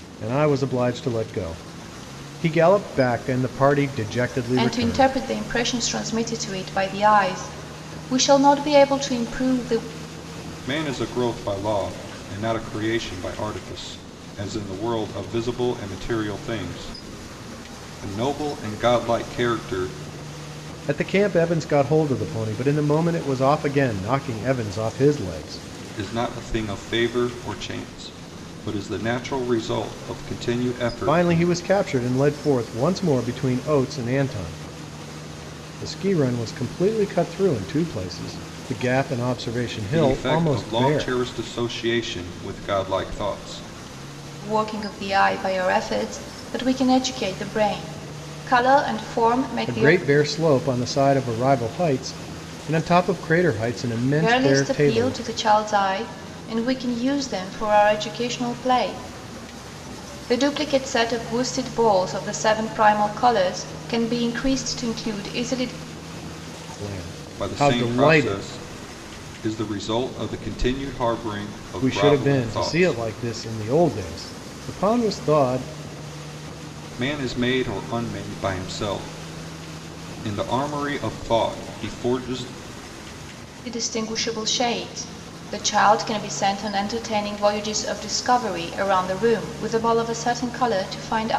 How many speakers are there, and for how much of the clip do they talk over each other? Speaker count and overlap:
three, about 7%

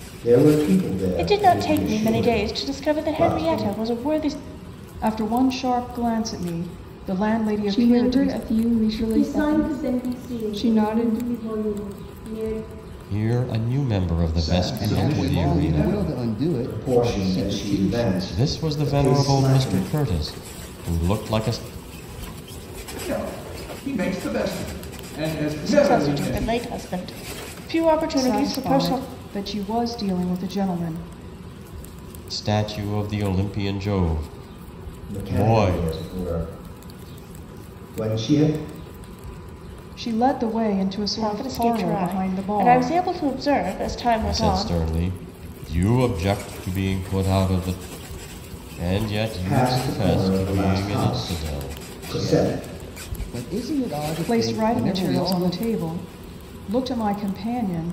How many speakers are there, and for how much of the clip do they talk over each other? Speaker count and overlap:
eight, about 35%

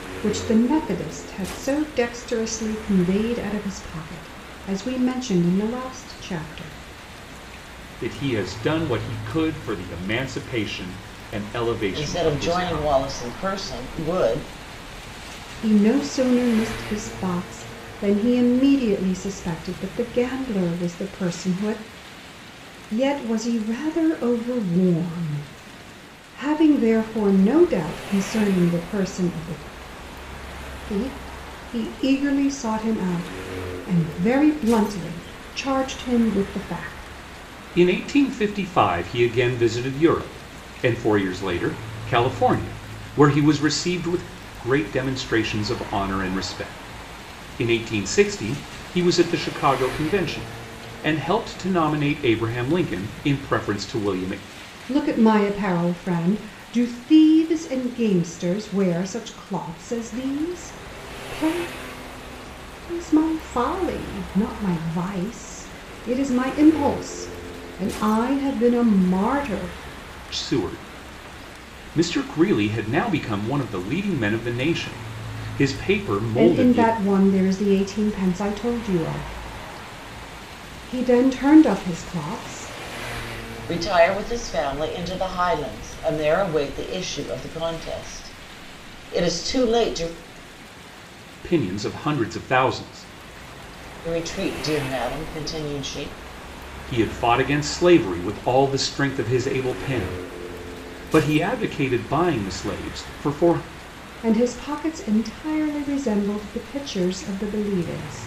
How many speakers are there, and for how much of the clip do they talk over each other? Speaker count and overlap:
three, about 2%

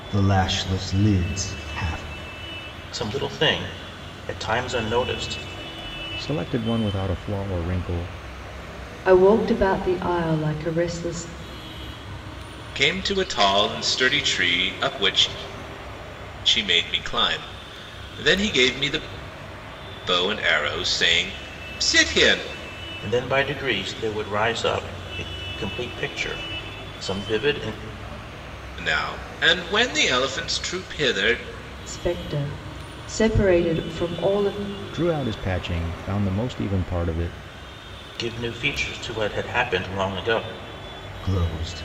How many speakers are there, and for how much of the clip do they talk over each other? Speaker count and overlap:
five, no overlap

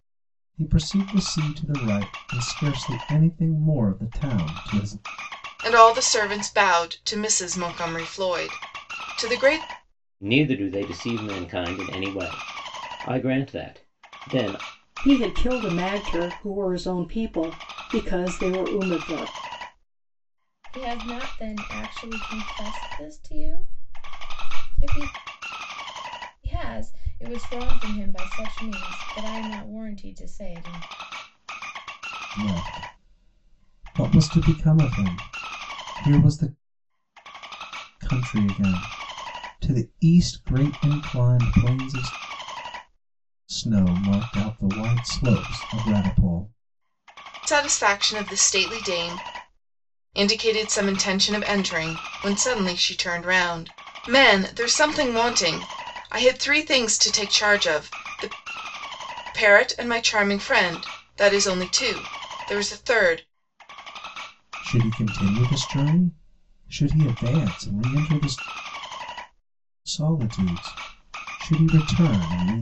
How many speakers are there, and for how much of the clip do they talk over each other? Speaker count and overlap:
five, no overlap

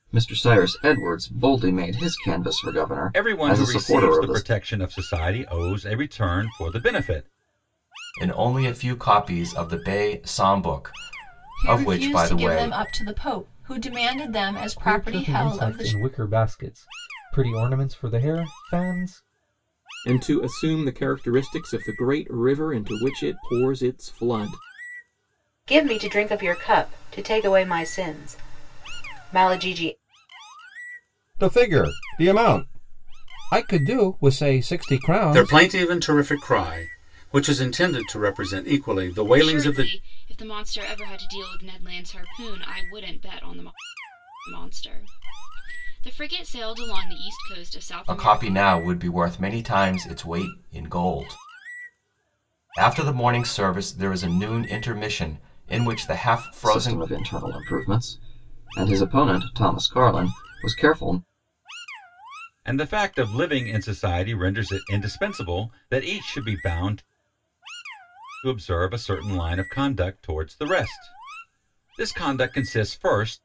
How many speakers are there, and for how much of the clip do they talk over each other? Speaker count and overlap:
ten, about 8%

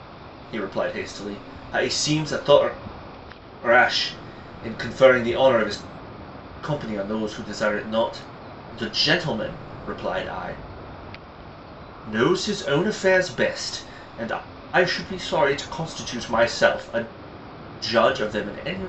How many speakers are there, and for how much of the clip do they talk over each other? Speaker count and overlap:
one, no overlap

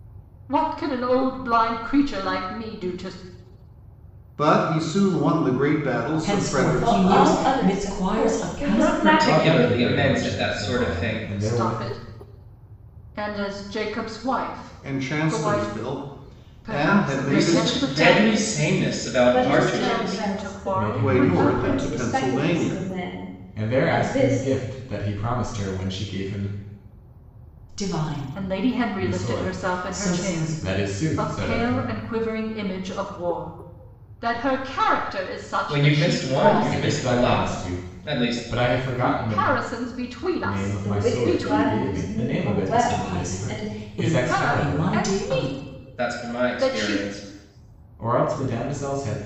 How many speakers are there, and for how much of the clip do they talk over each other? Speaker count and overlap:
six, about 55%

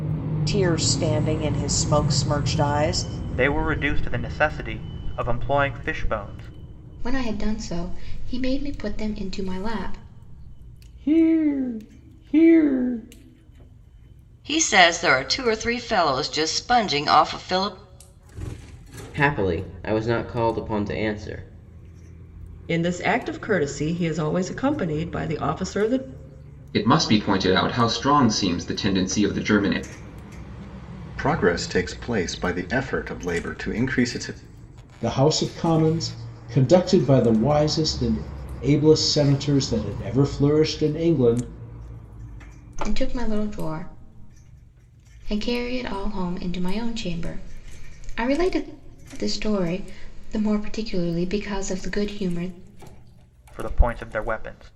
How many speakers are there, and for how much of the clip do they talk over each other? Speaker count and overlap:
ten, no overlap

